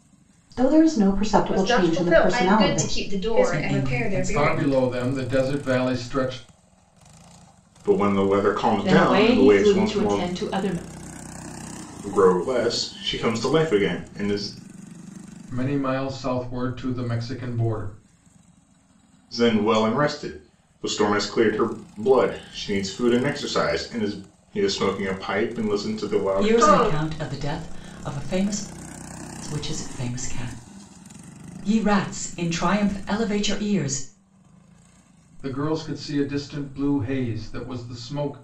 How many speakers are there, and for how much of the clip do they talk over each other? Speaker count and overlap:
7, about 14%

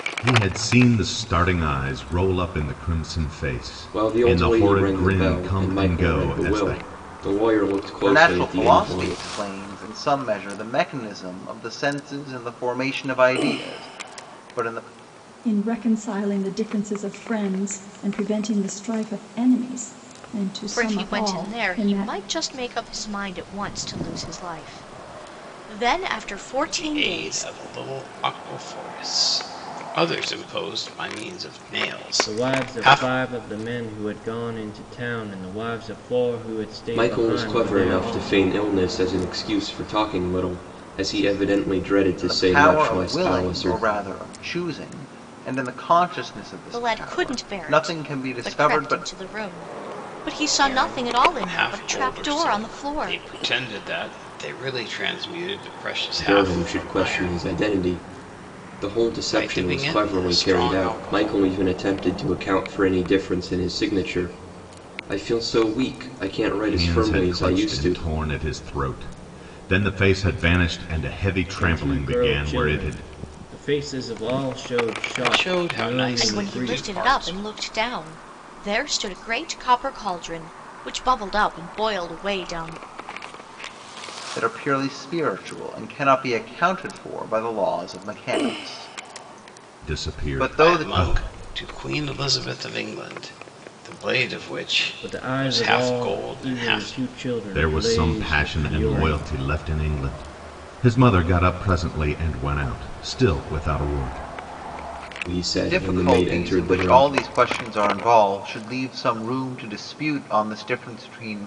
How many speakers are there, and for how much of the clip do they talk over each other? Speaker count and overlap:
7, about 28%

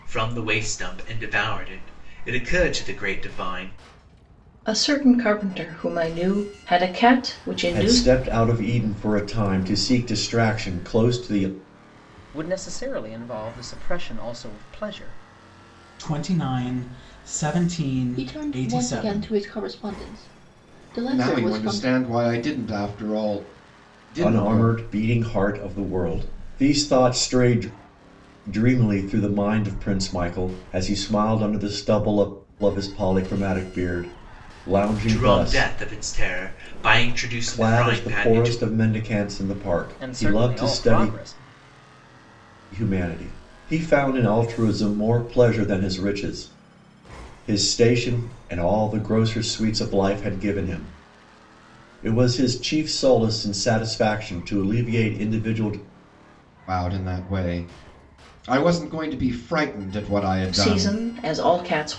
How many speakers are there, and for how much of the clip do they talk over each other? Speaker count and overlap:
7, about 10%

